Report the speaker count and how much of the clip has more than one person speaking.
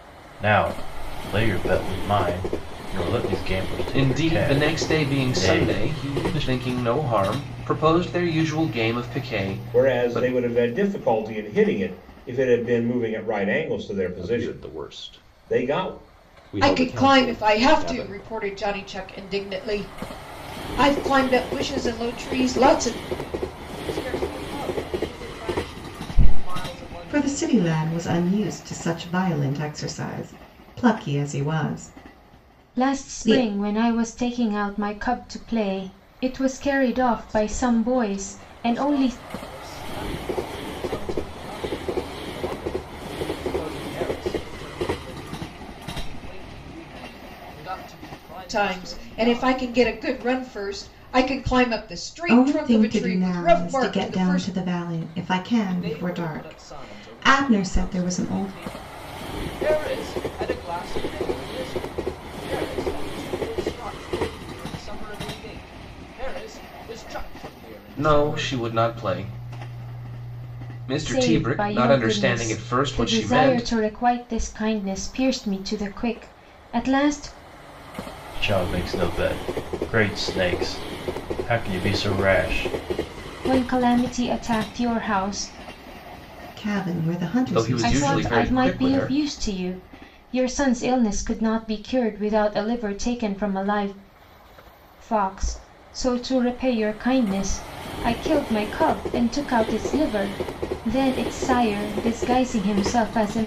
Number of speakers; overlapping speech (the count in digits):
8, about 23%